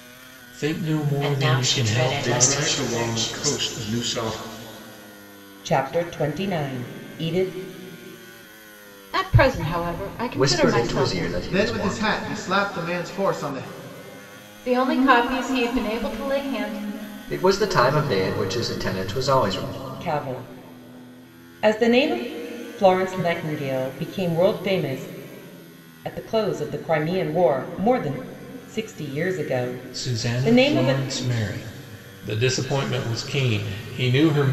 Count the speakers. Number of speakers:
eight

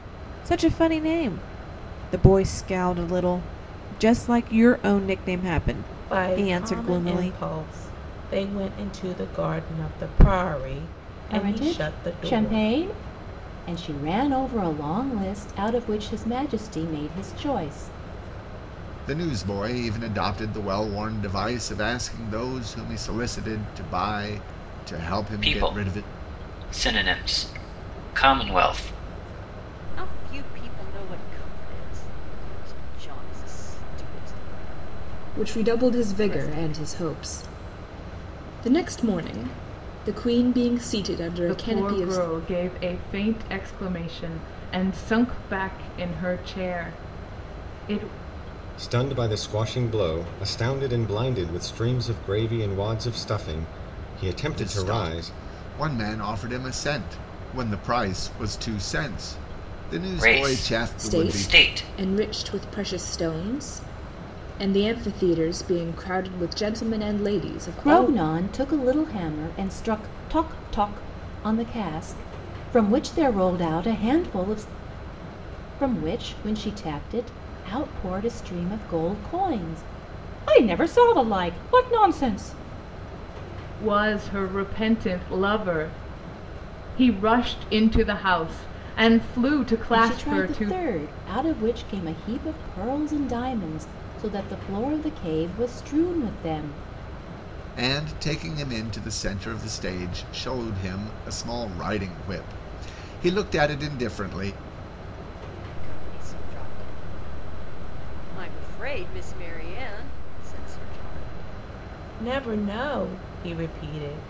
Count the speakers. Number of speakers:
nine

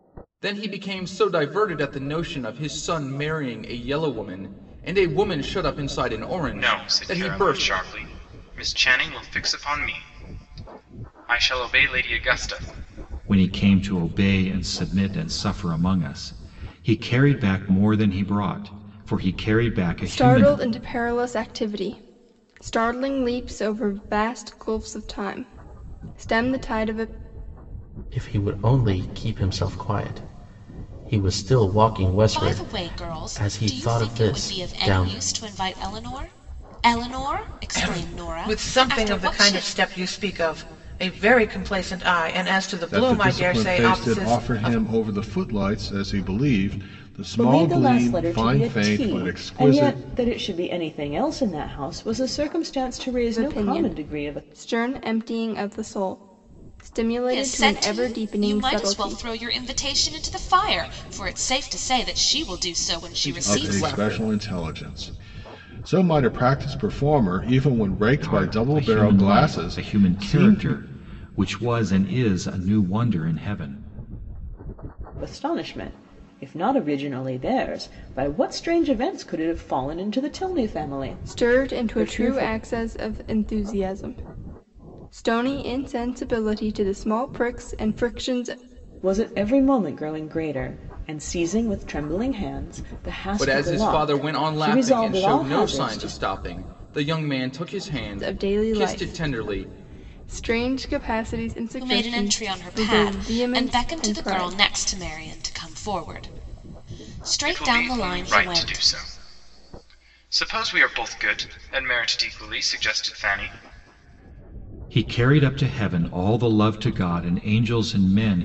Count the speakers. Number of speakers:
nine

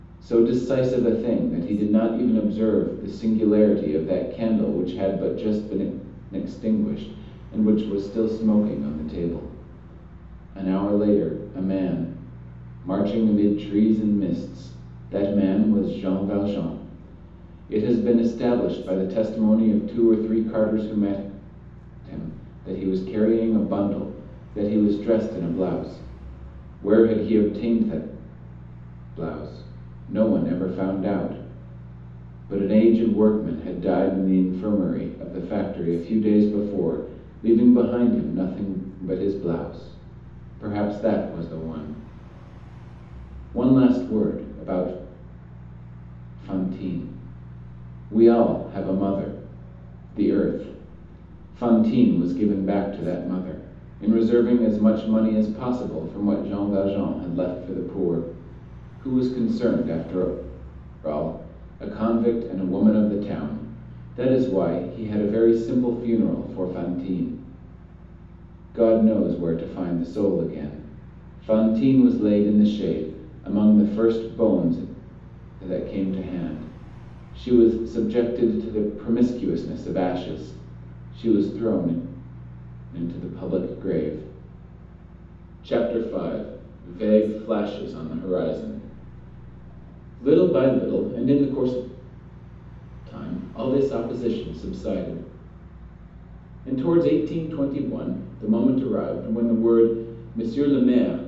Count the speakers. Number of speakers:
one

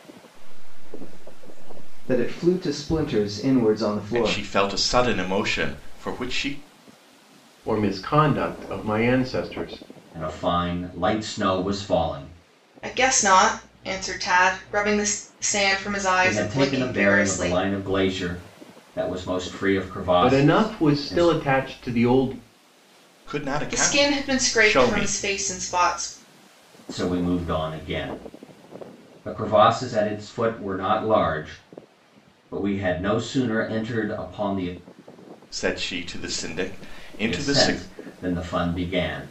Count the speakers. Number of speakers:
six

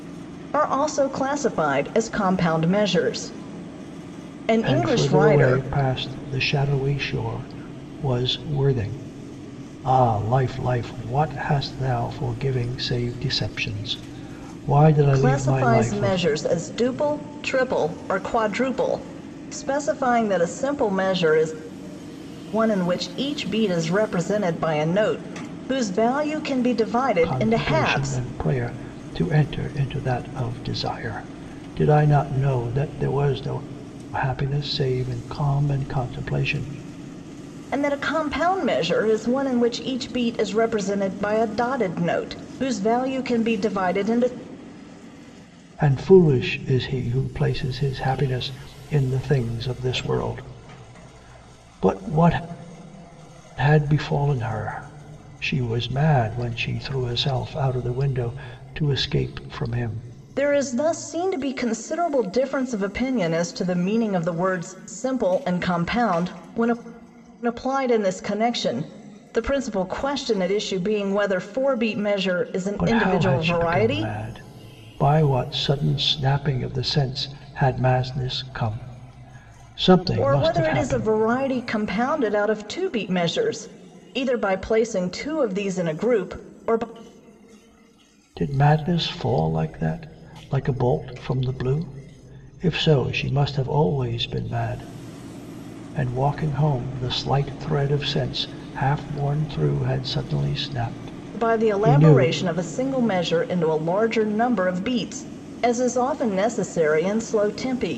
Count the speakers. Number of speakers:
two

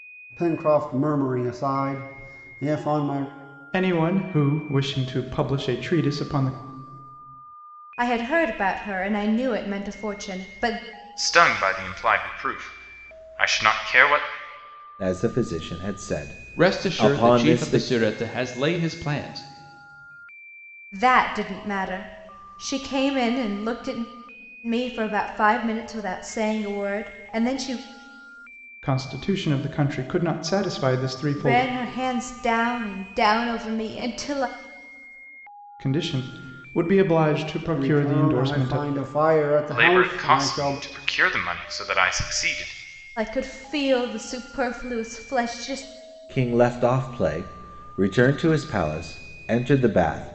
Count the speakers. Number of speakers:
six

